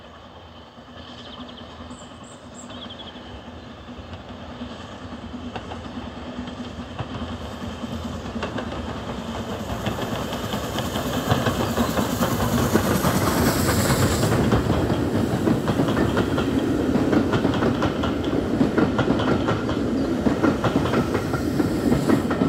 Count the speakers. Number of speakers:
0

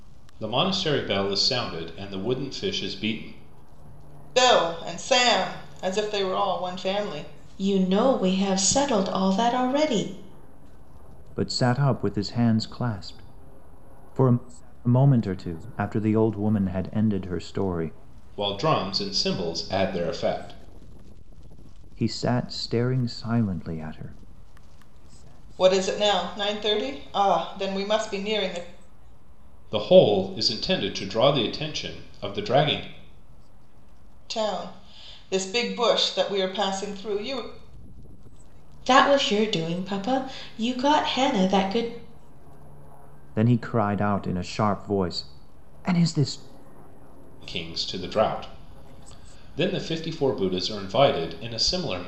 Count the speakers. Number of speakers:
4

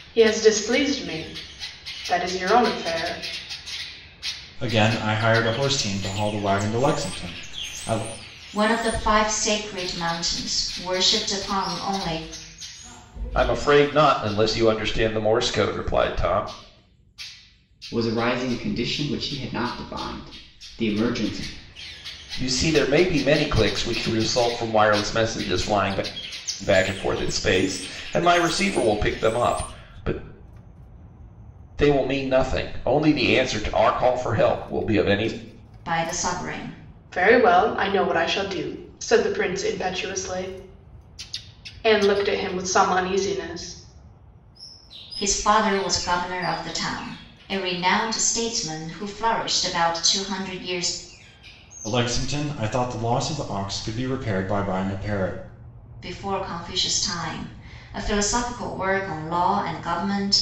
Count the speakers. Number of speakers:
5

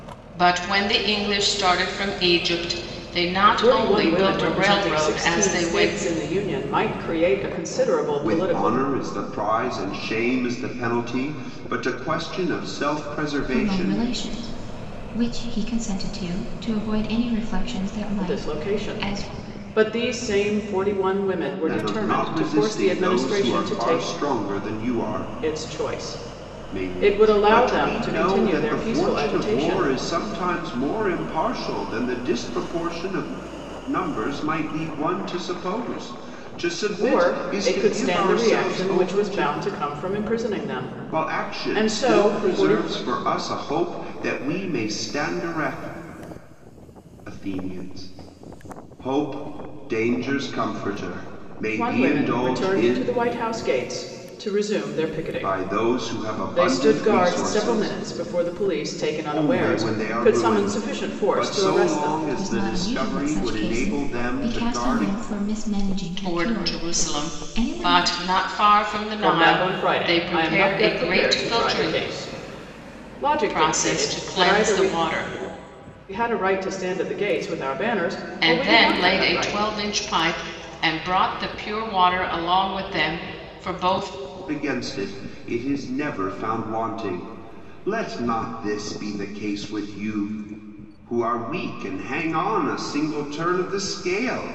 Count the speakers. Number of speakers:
4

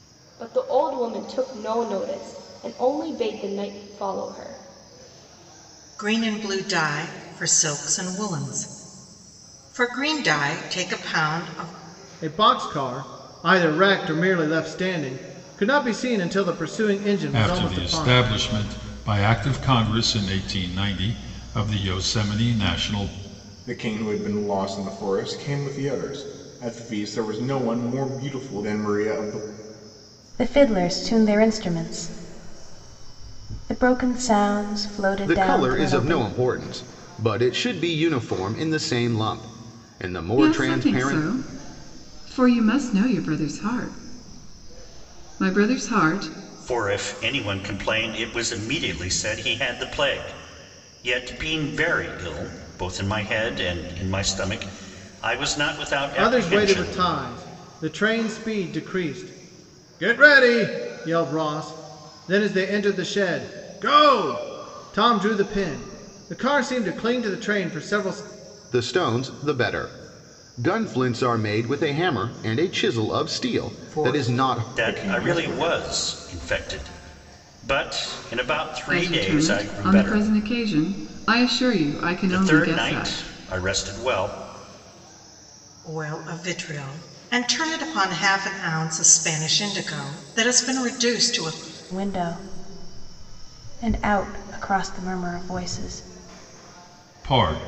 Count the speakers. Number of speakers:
9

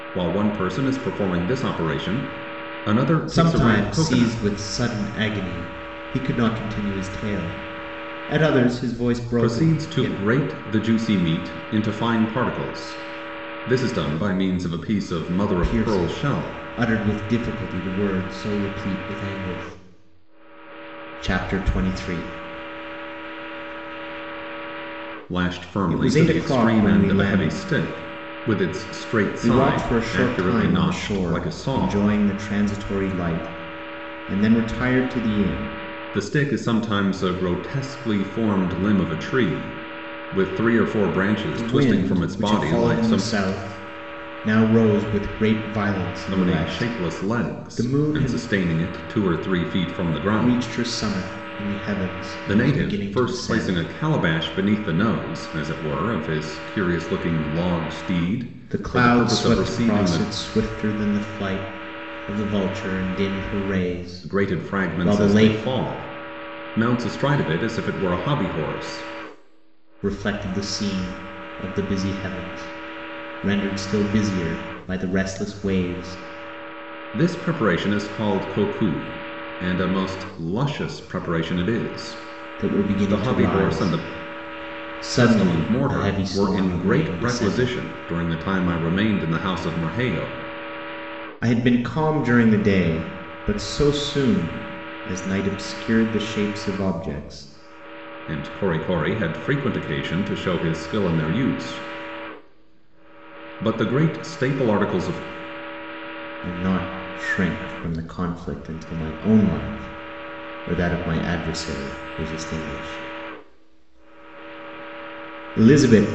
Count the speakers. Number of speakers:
2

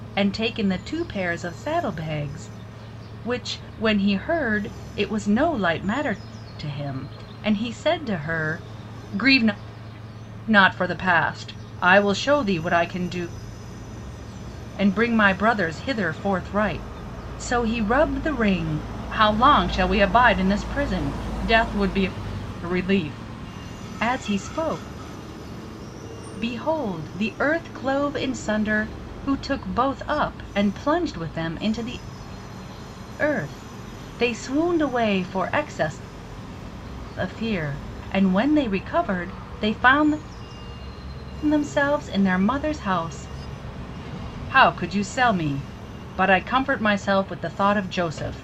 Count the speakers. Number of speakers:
1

